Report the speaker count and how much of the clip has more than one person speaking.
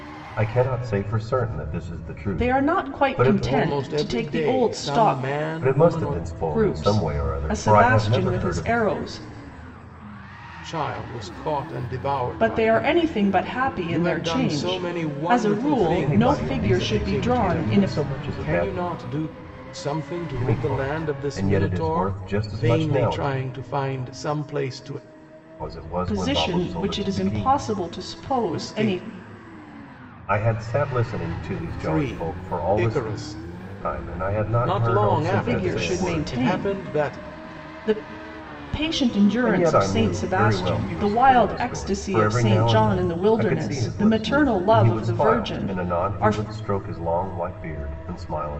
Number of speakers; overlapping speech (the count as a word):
three, about 55%